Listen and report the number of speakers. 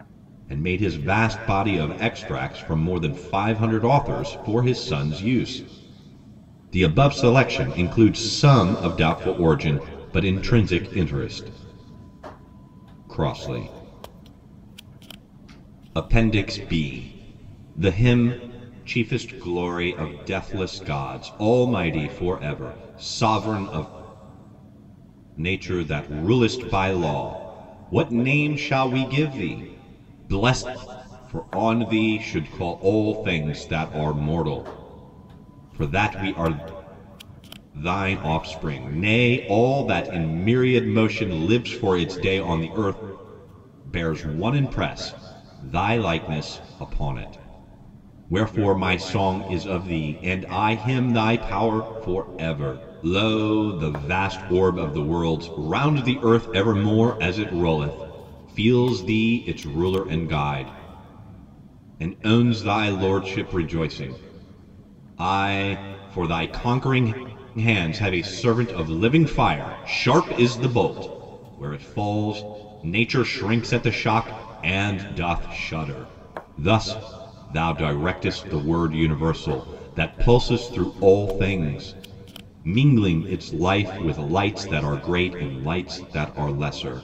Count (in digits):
1